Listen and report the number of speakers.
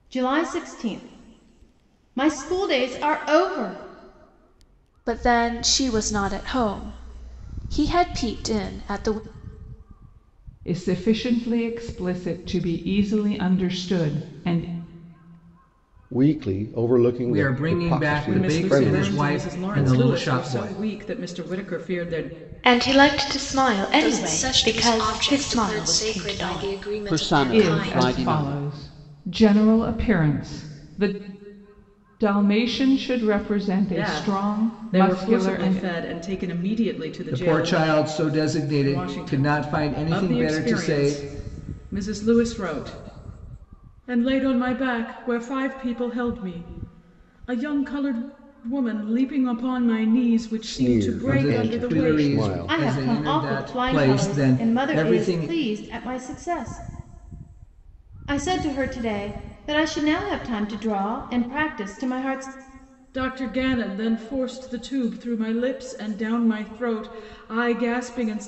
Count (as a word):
nine